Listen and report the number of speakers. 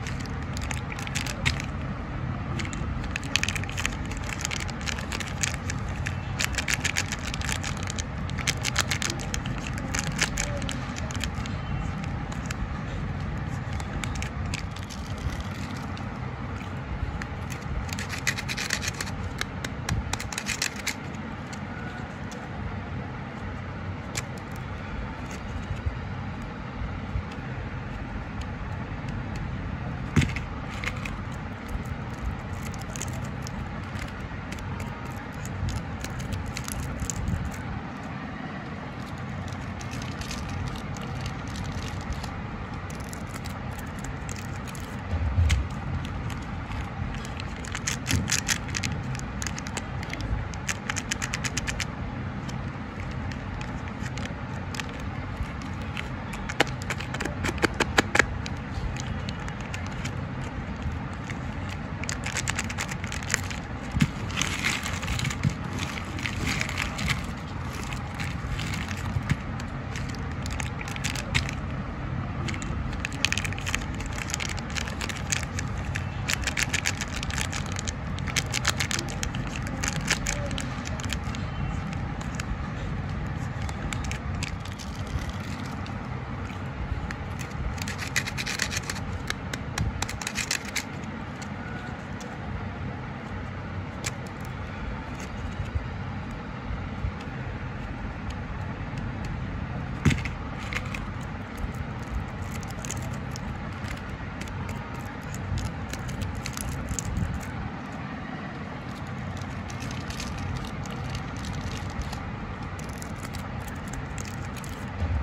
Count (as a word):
zero